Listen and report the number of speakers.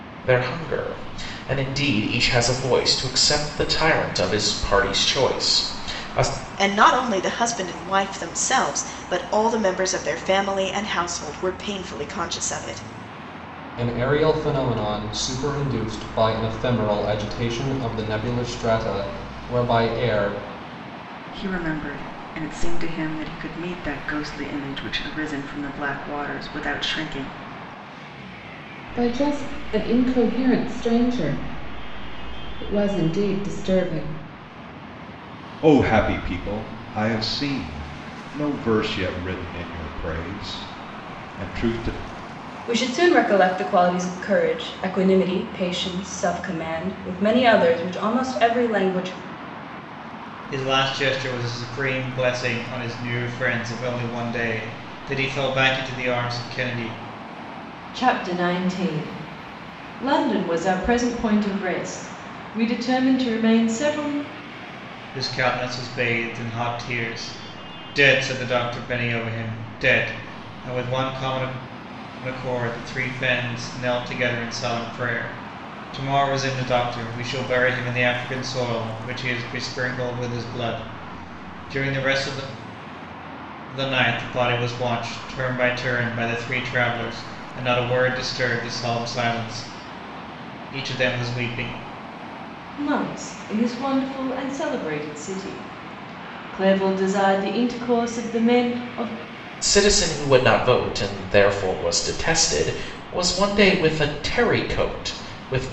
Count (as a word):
nine